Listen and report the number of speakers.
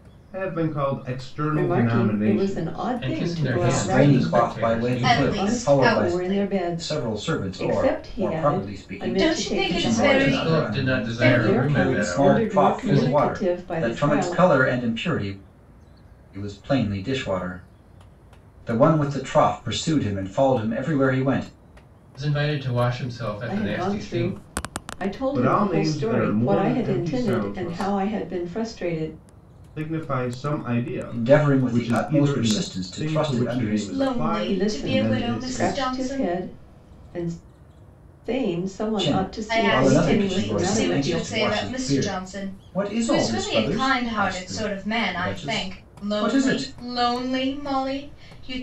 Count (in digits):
5